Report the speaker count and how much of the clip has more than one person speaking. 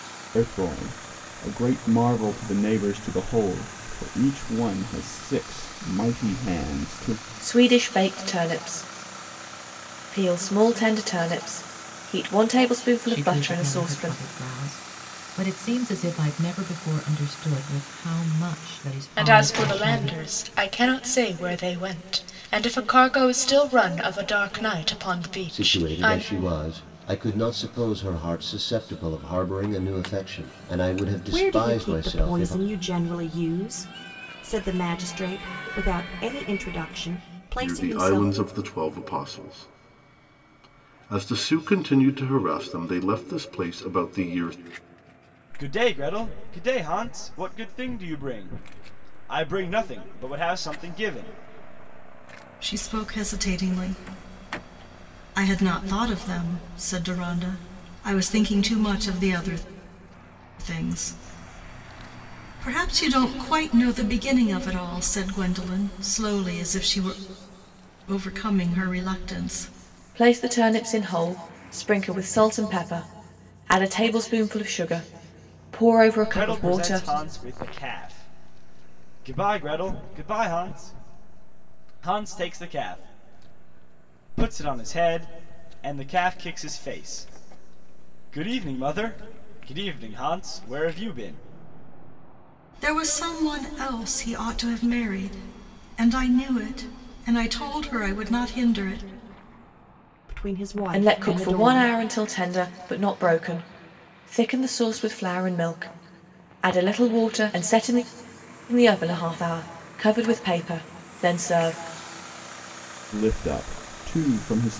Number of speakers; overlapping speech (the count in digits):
9, about 6%